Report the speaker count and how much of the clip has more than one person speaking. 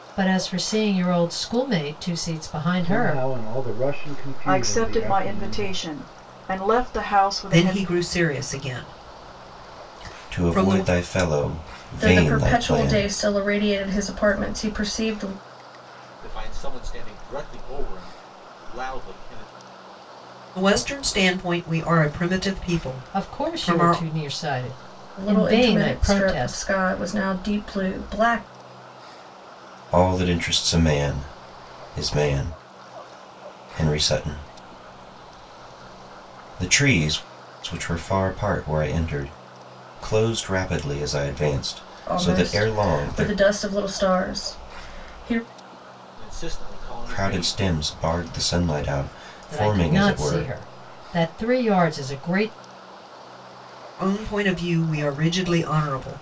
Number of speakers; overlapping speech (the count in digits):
7, about 17%